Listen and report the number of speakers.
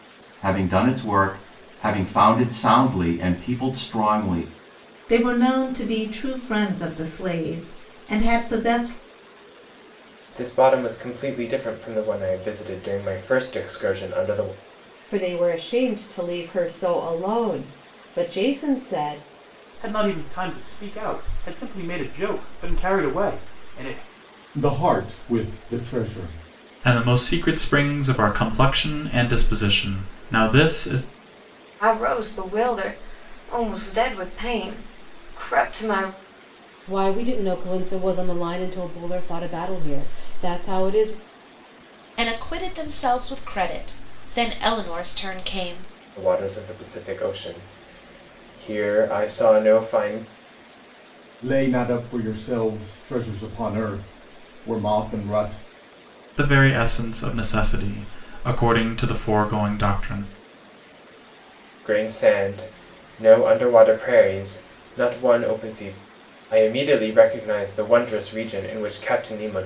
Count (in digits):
10